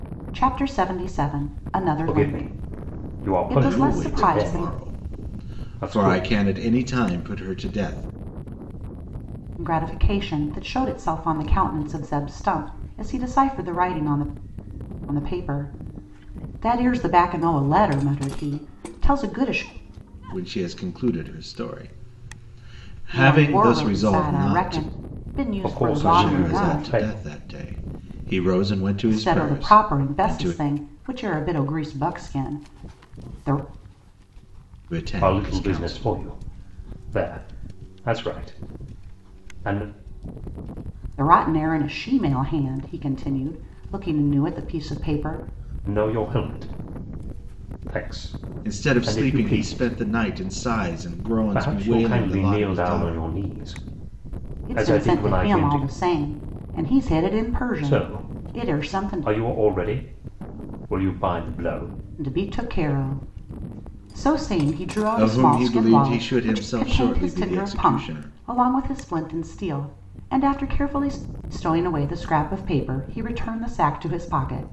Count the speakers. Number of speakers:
three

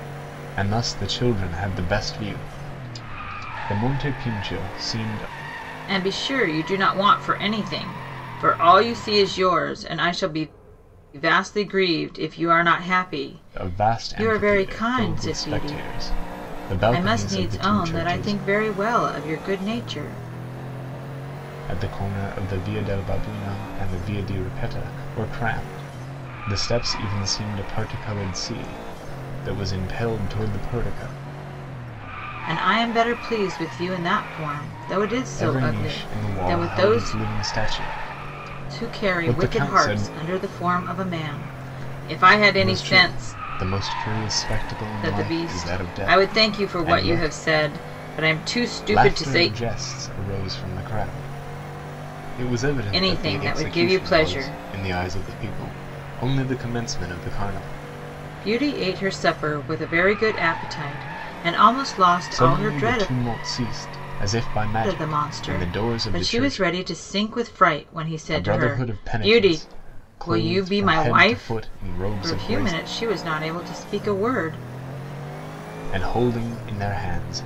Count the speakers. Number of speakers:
two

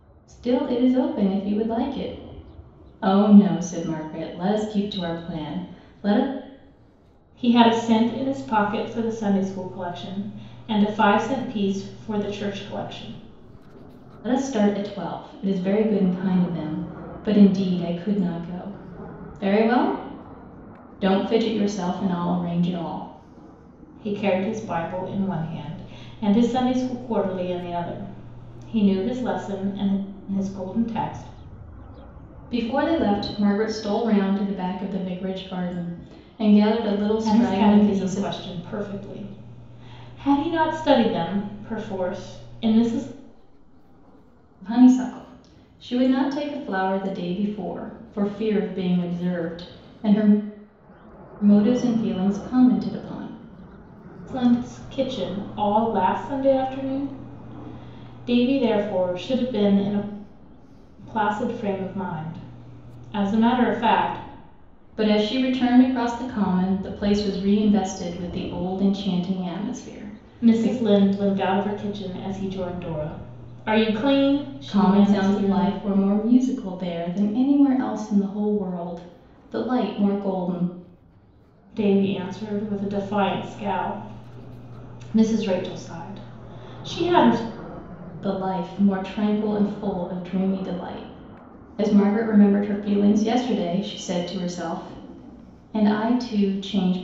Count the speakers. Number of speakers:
two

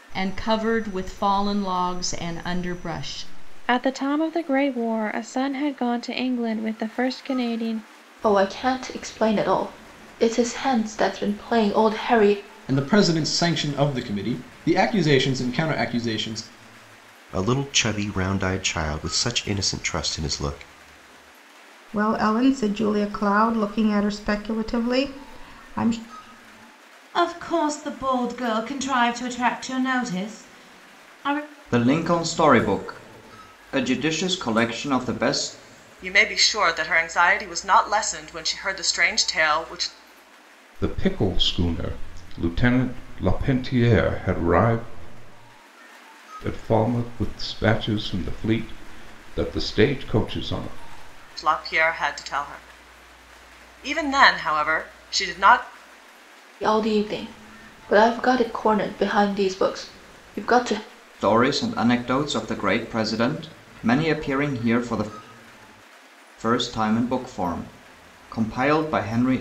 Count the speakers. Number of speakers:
ten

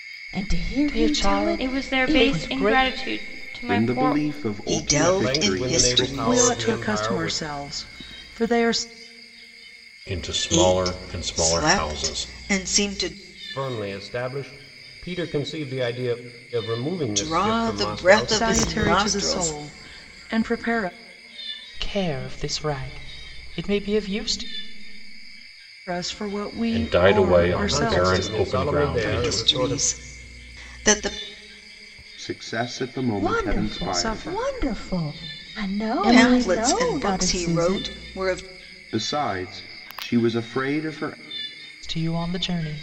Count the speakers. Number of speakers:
eight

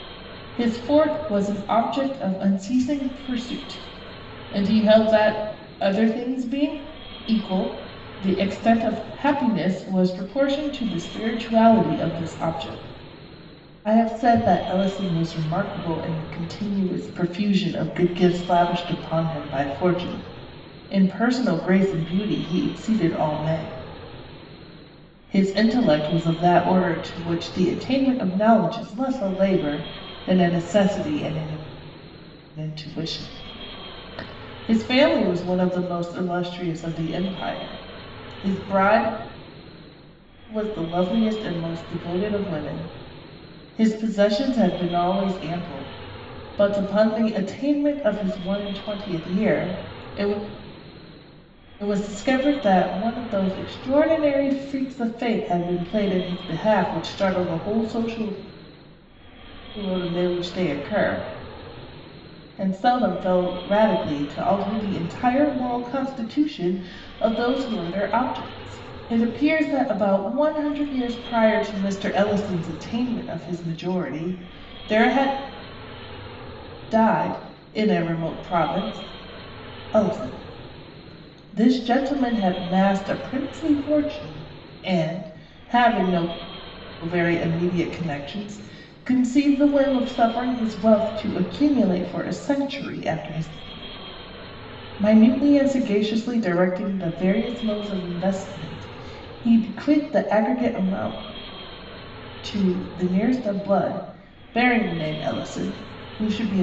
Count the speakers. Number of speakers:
one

